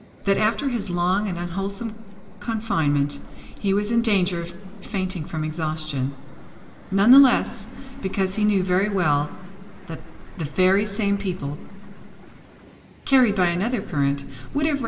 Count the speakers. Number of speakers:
one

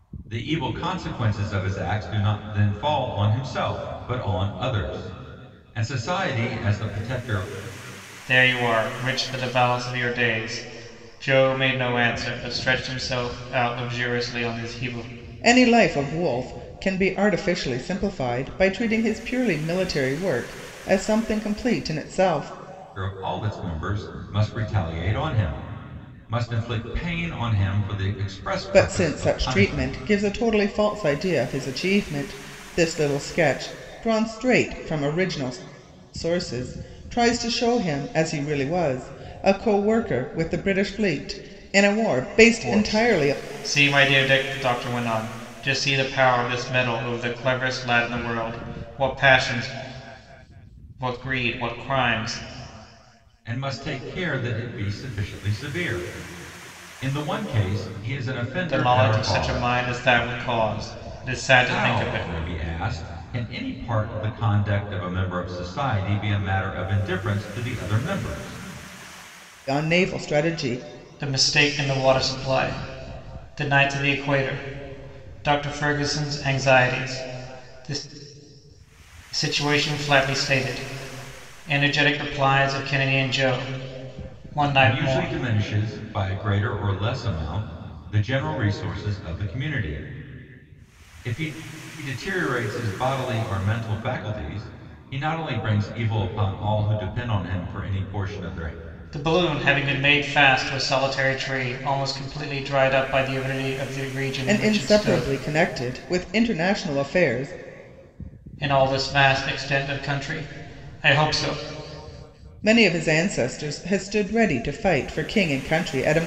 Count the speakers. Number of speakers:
three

